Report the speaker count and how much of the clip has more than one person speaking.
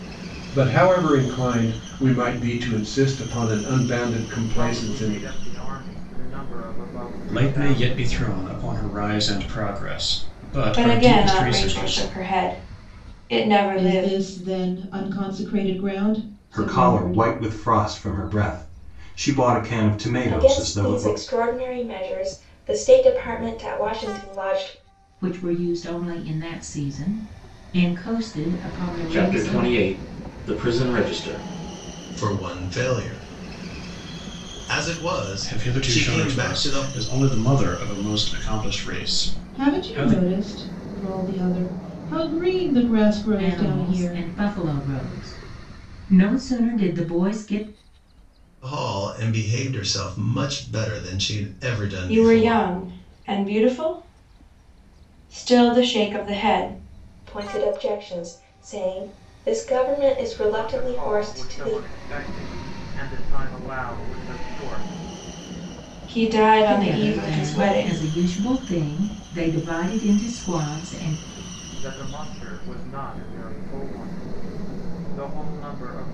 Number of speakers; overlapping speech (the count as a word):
ten, about 17%